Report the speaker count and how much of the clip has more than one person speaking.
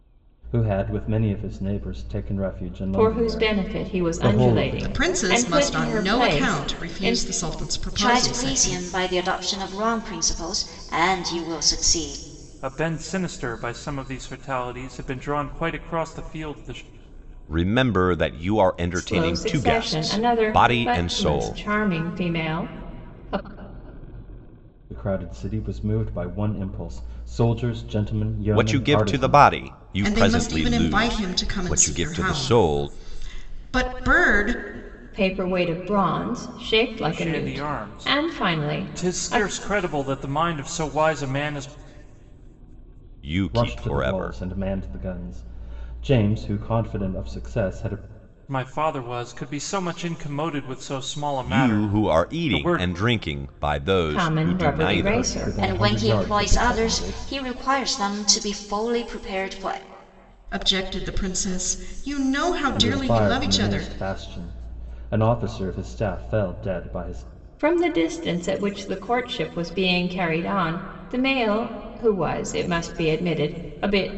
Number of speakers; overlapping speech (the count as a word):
six, about 29%